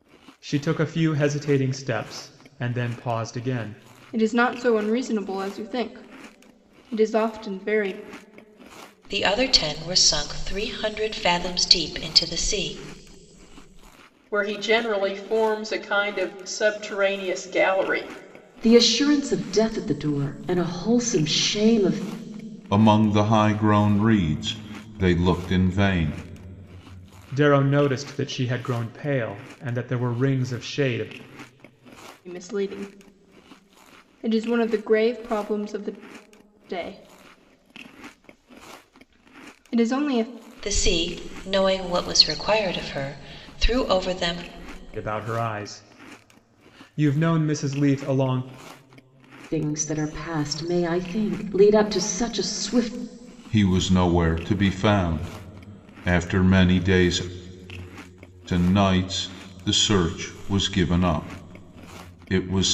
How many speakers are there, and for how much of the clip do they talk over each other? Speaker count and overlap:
6, no overlap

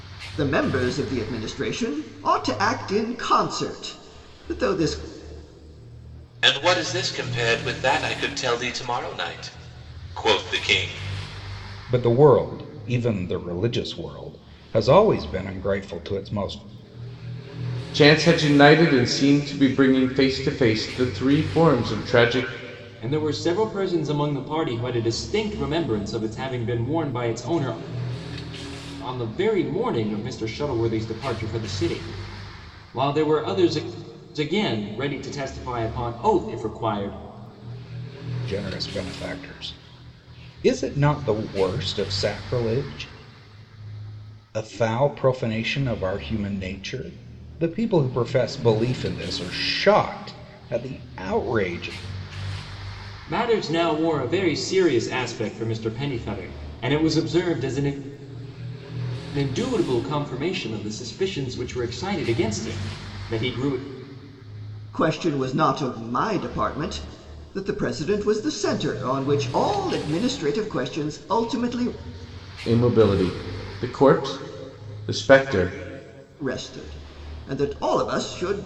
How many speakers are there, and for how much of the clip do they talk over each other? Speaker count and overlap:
5, no overlap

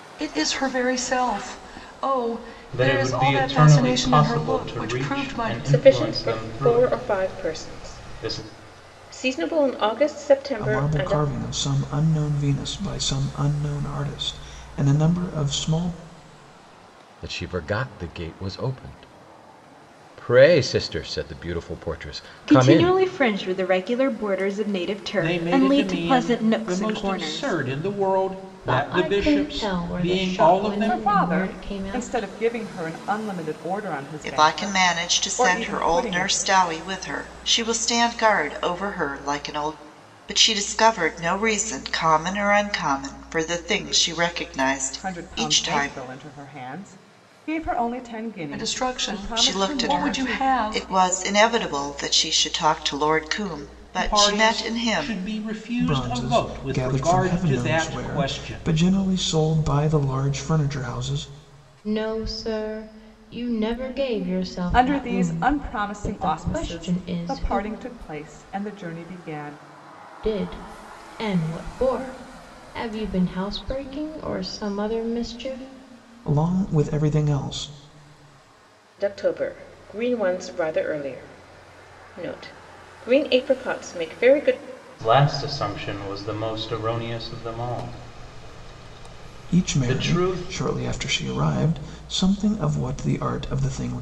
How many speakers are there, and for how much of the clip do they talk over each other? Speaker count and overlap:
10, about 29%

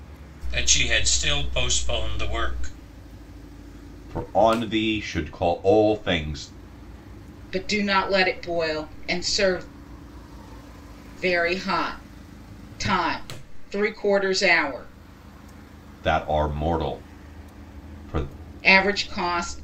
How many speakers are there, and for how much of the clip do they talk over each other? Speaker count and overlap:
3, no overlap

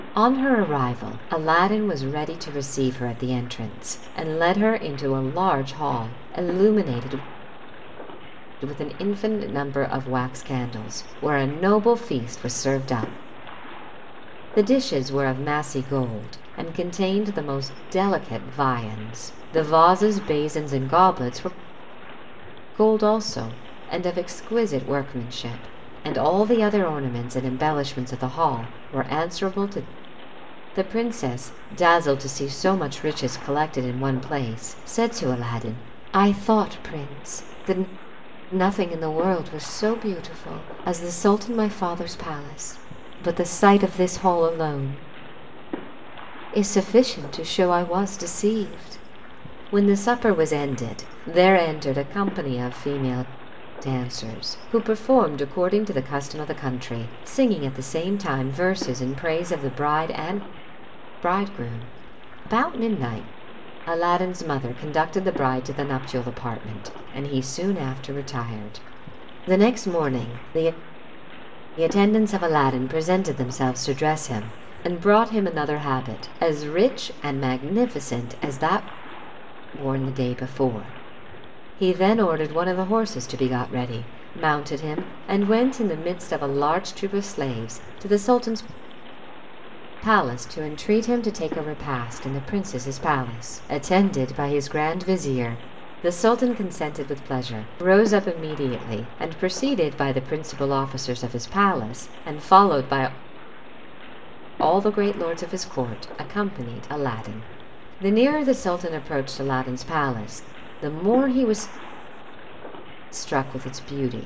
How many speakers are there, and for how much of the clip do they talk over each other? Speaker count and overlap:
1, no overlap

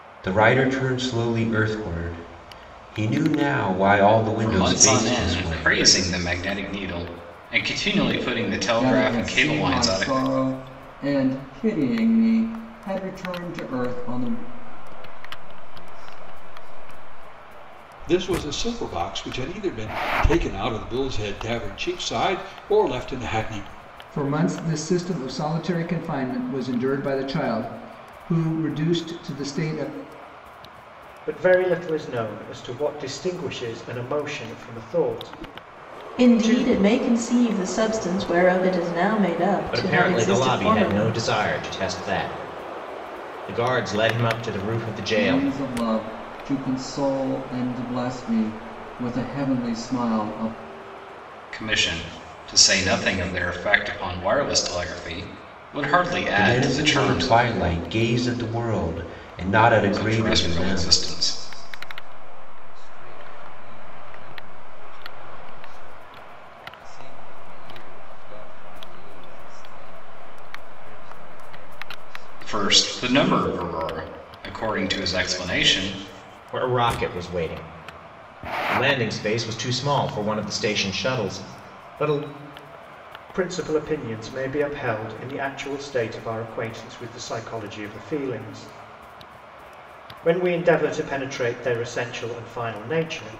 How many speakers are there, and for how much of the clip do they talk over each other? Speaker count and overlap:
9, about 9%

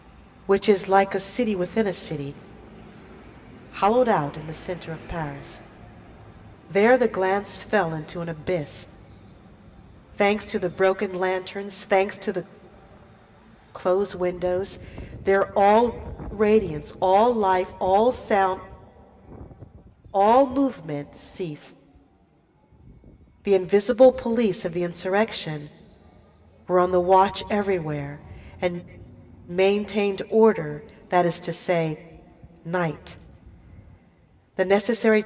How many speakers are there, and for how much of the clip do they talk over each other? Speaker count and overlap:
1, no overlap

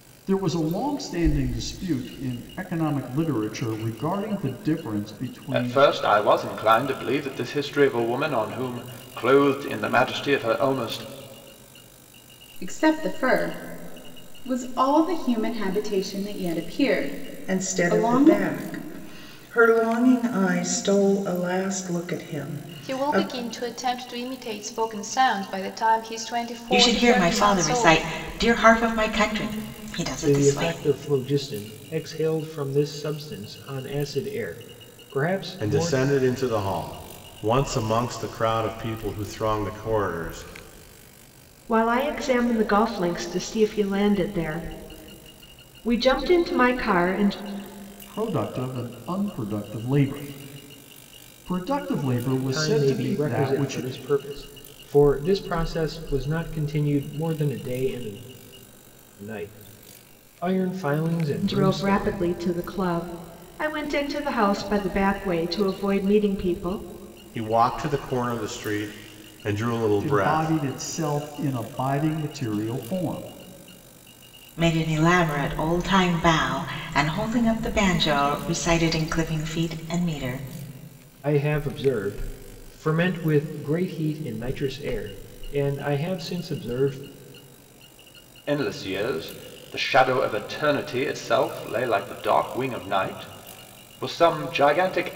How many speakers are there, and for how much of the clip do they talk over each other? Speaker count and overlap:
9, about 8%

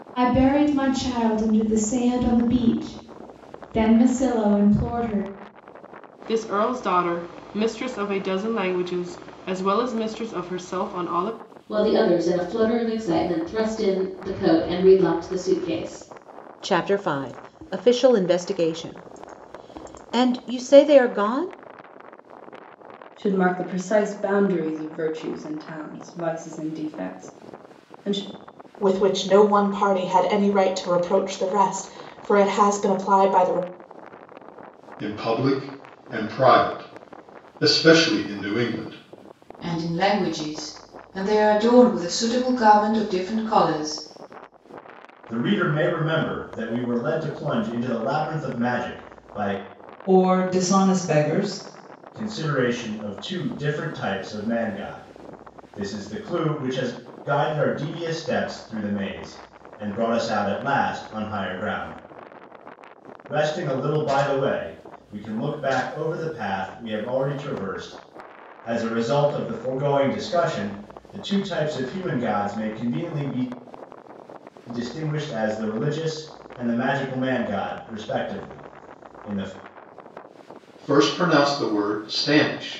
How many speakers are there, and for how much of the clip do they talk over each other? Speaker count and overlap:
10, no overlap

